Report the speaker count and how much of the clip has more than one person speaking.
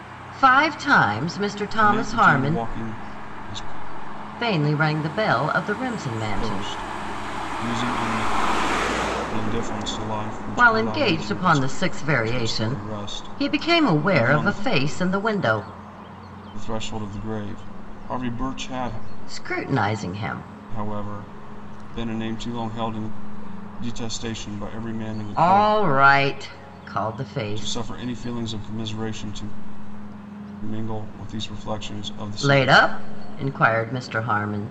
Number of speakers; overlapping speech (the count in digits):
2, about 16%